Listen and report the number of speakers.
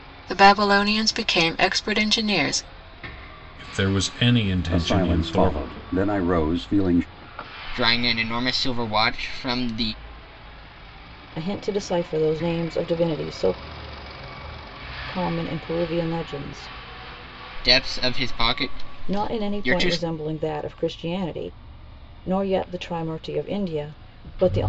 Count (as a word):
five